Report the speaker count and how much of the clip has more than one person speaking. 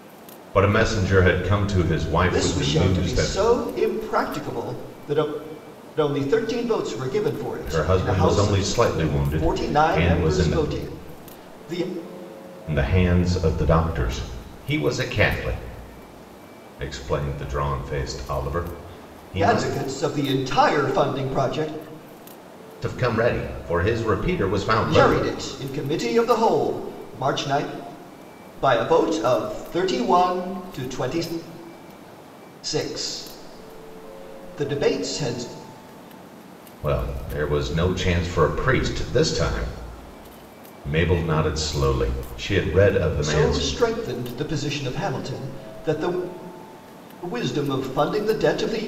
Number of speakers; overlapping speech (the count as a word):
two, about 10%